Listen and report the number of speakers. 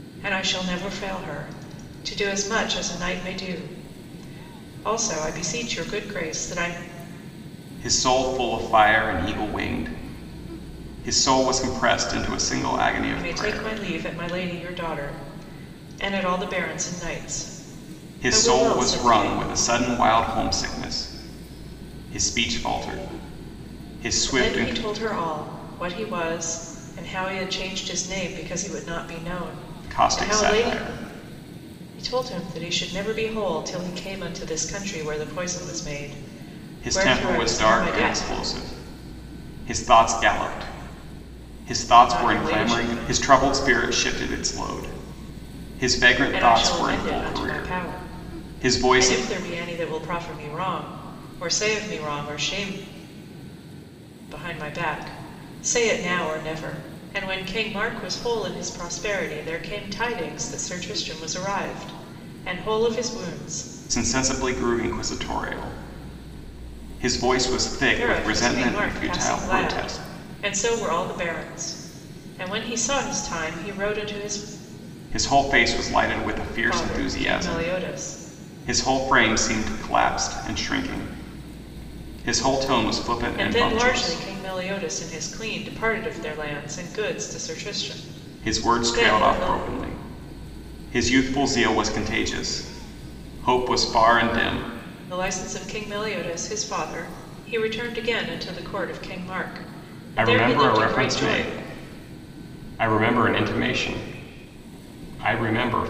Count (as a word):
two